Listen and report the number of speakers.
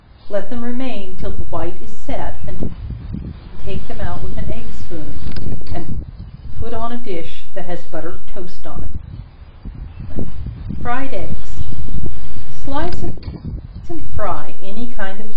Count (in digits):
1